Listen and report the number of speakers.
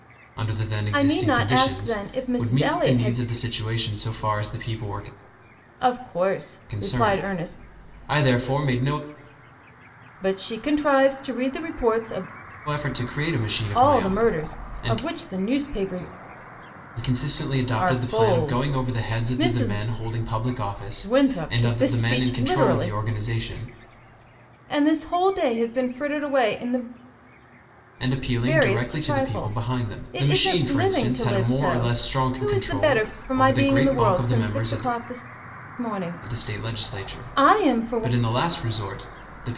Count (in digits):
2